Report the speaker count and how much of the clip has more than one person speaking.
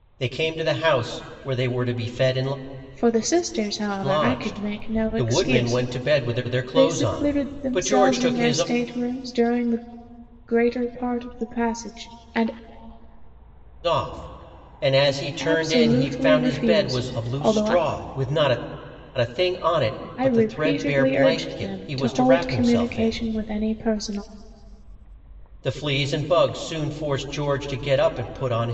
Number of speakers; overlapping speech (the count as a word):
two, about 35%